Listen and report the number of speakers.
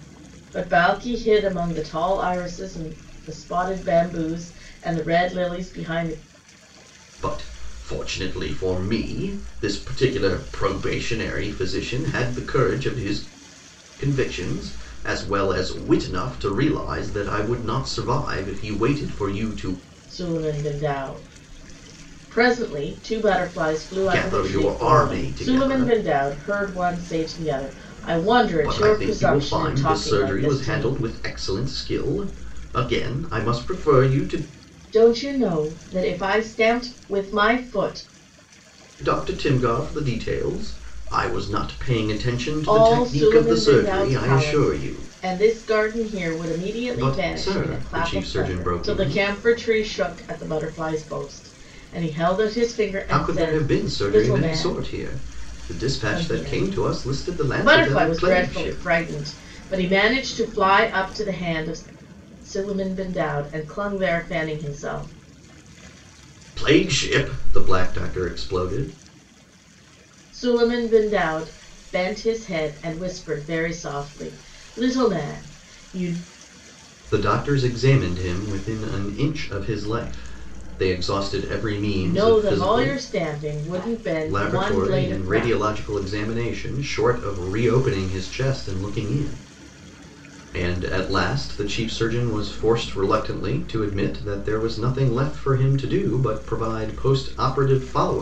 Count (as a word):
two